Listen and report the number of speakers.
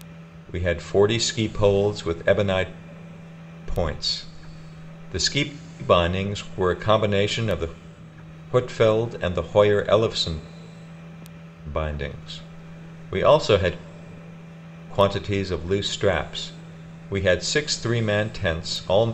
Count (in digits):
1